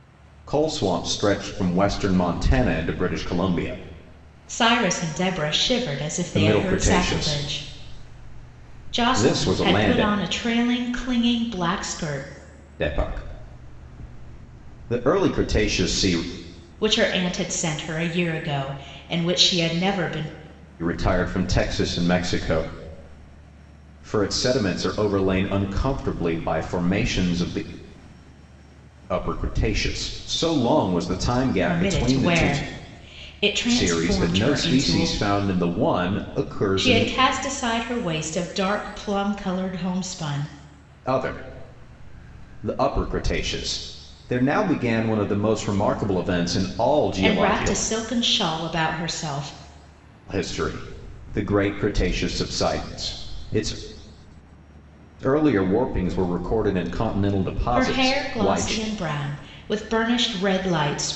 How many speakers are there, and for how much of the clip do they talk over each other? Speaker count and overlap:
2, about 12%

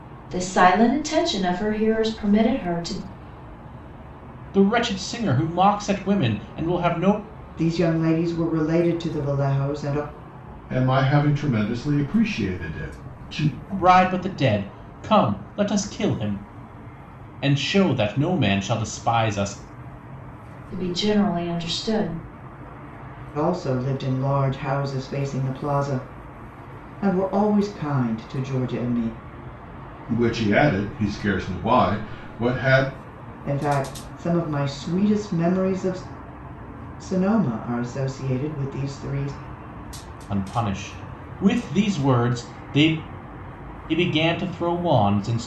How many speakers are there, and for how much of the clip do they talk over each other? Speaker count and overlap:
4, no overlap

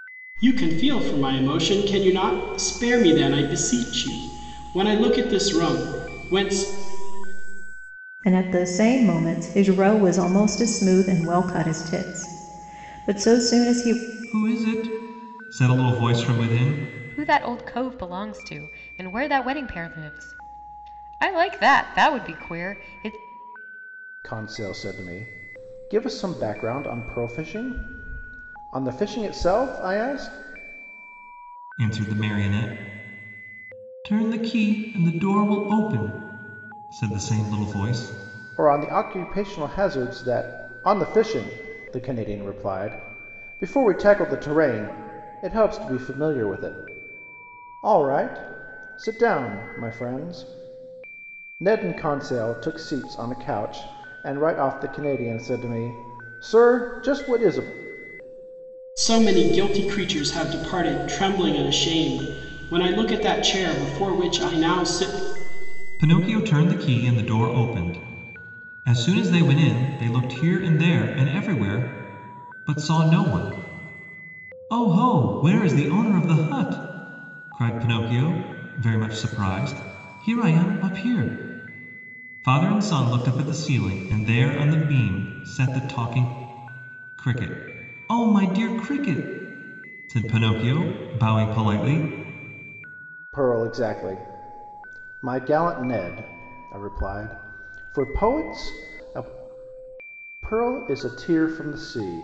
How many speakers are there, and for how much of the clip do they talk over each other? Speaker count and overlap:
5, no overlap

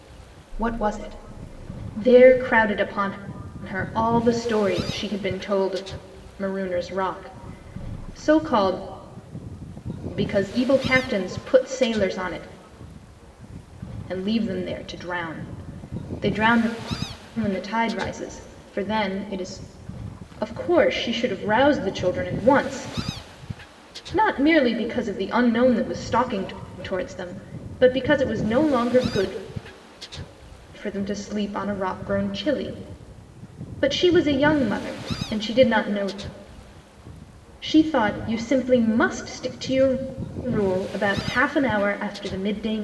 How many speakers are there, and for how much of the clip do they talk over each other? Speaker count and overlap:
1, no overlap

